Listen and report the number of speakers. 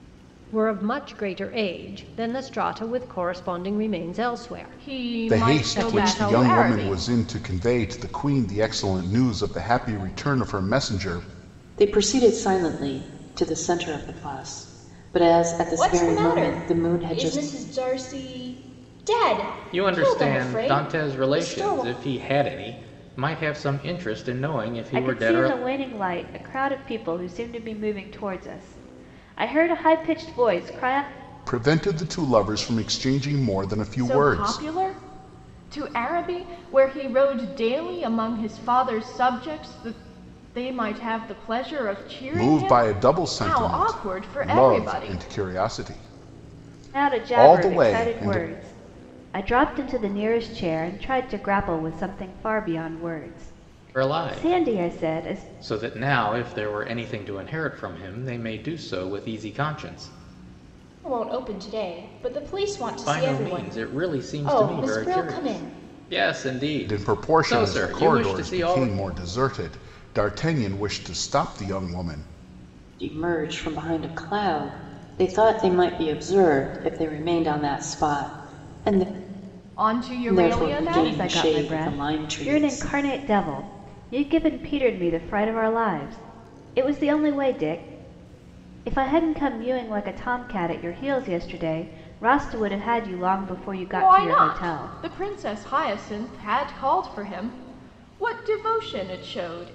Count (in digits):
7